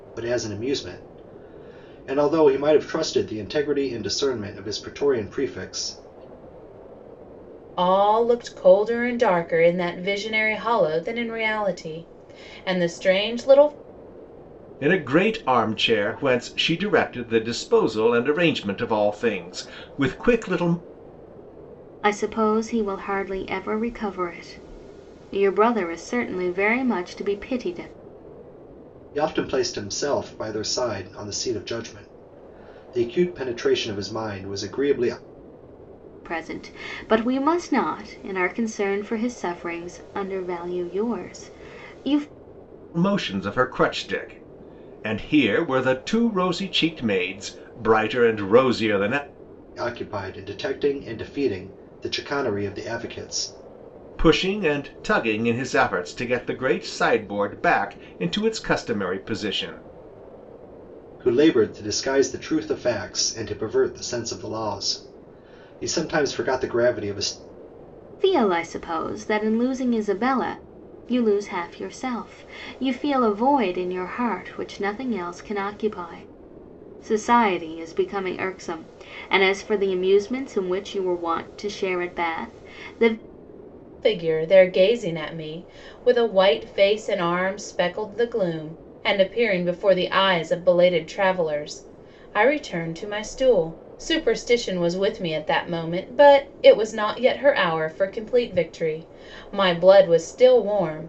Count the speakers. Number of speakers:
4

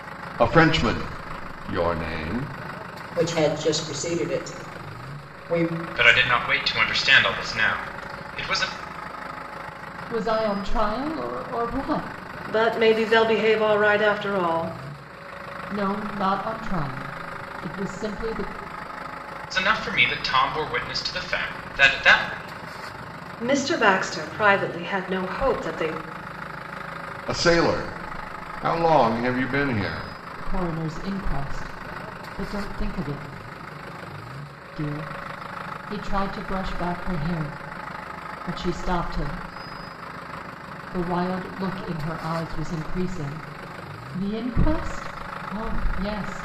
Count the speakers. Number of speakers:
5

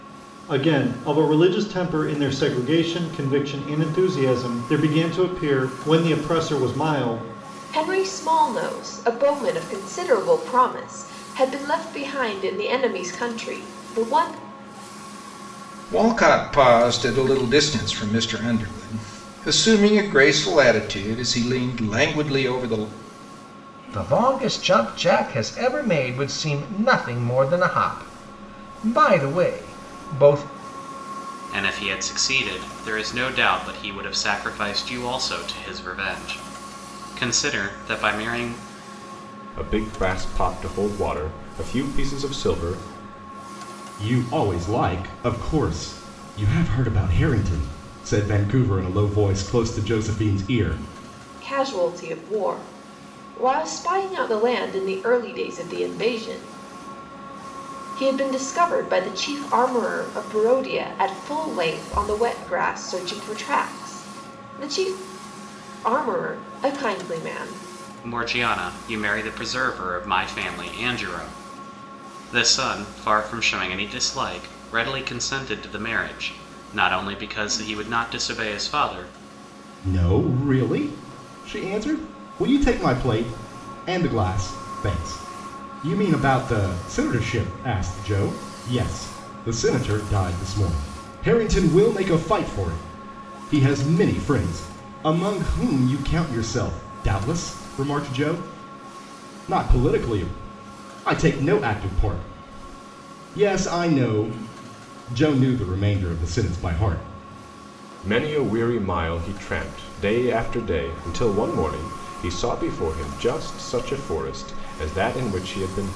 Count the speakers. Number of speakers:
7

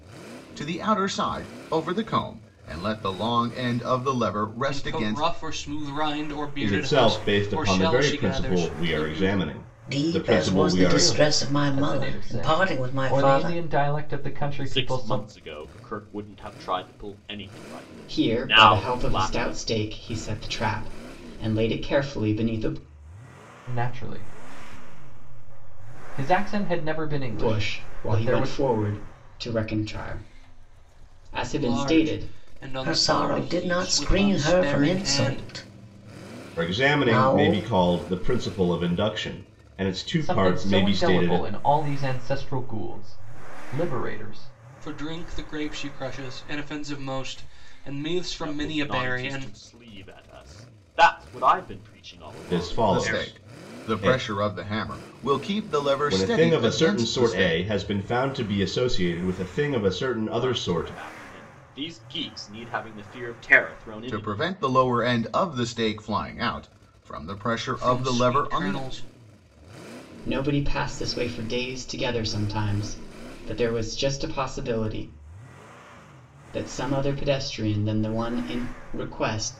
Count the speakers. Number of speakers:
7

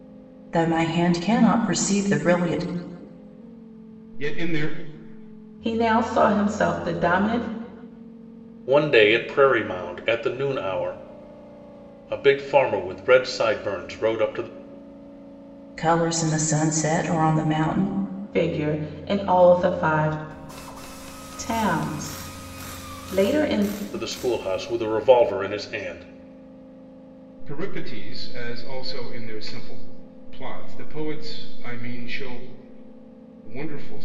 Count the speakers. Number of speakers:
4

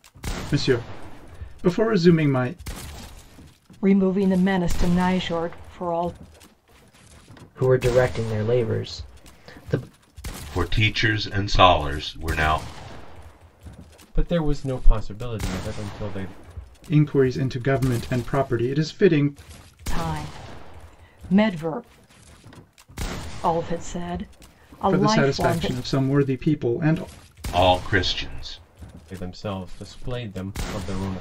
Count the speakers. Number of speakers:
5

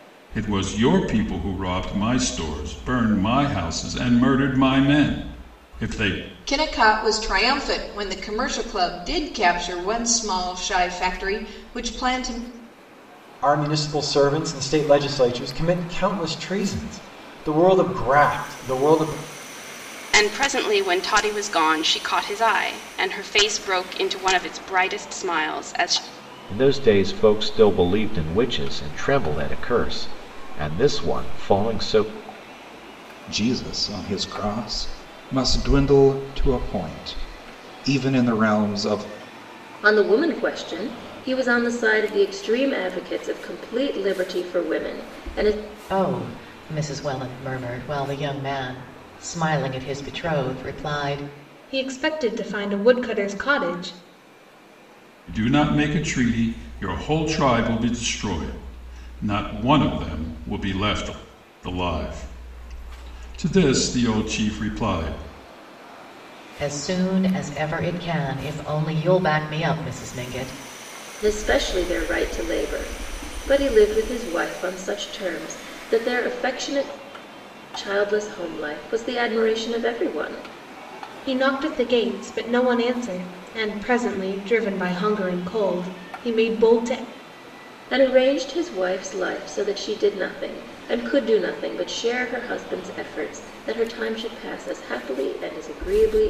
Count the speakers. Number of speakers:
9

